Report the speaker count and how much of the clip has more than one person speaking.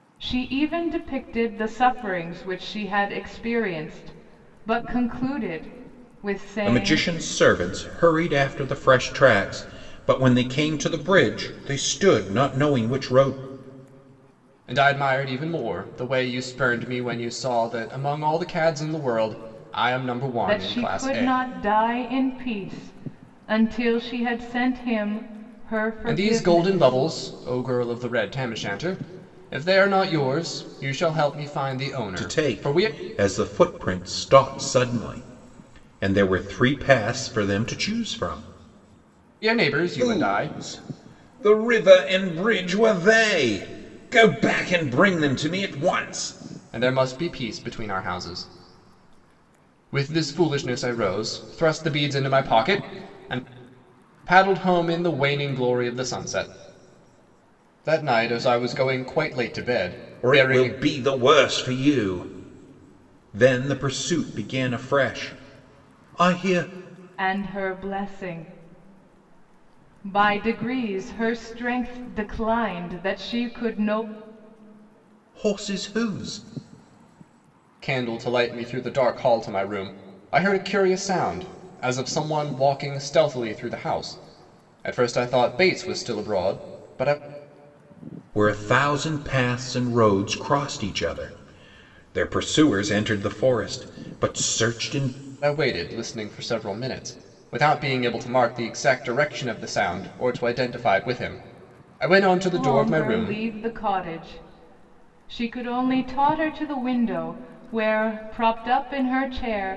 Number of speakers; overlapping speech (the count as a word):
three, about 5%